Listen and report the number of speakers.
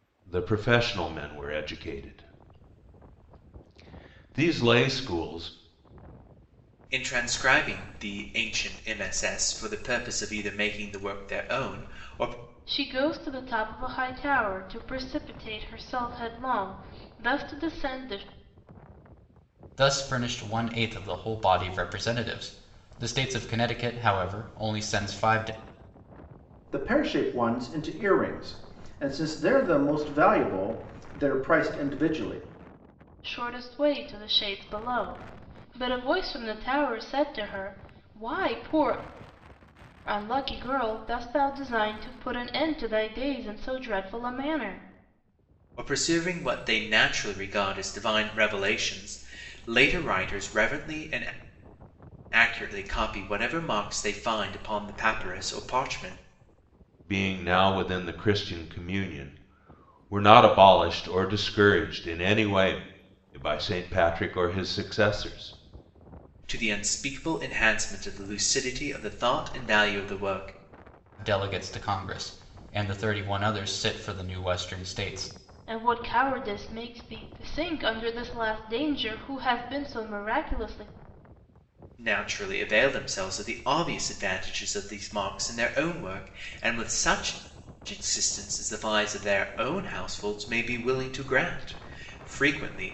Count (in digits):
5